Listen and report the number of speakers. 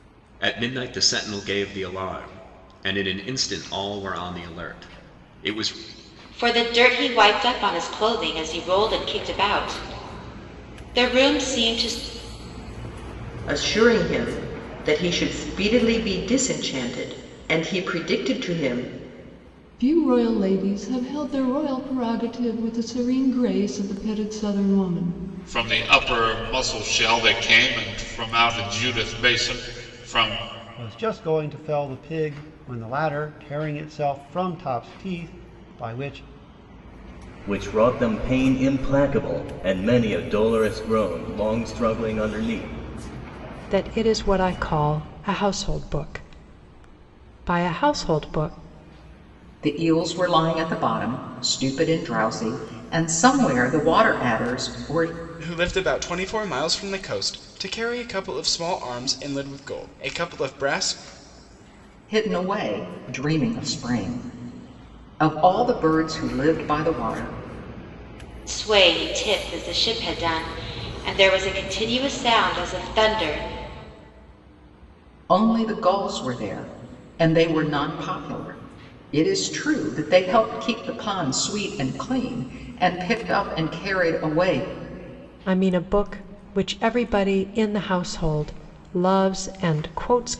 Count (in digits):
10